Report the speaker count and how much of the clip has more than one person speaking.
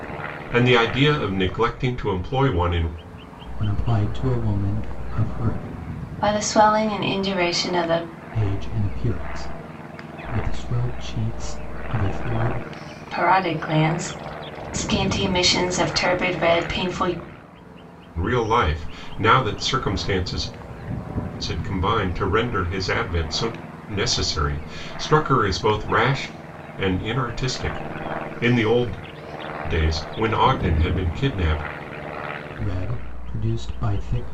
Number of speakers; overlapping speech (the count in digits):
3, no overlap